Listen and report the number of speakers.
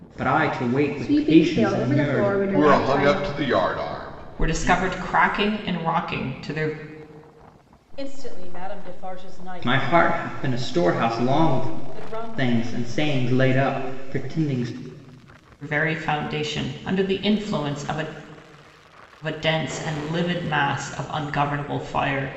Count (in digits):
5